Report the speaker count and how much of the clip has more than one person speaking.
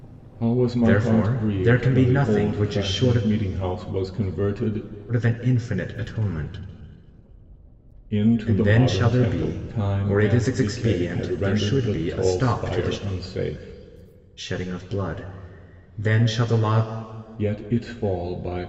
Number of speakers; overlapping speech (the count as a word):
two, about 38%